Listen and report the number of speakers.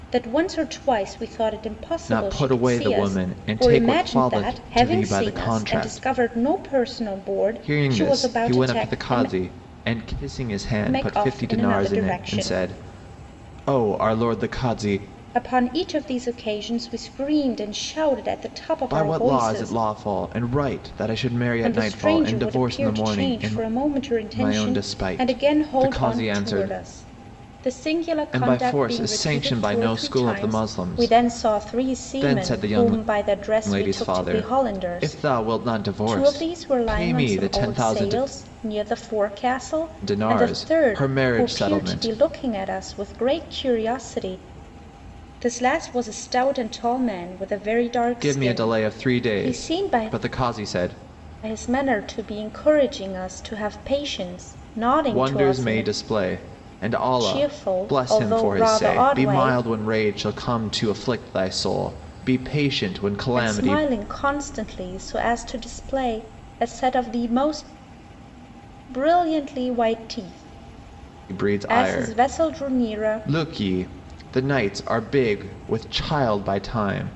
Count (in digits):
2